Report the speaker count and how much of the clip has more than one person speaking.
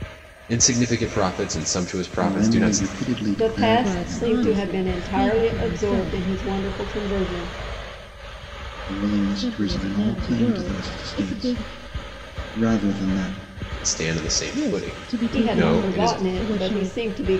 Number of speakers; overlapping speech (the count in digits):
4, about 49%